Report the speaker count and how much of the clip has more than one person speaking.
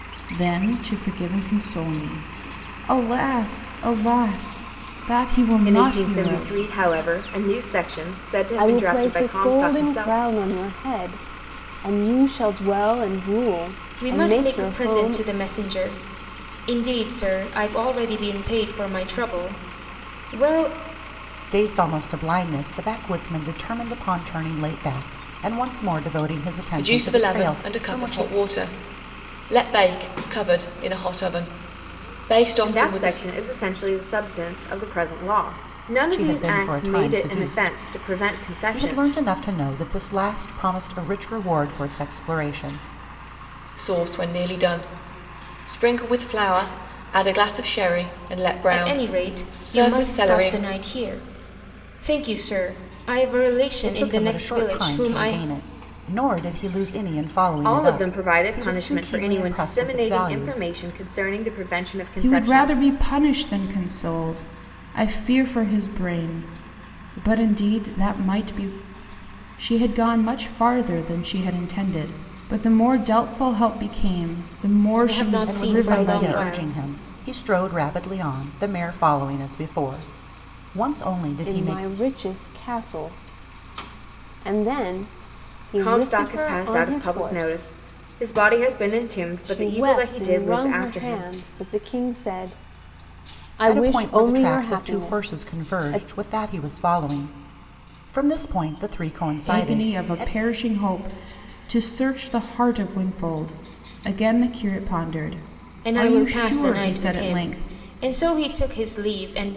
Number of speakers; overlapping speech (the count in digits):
6, about 25%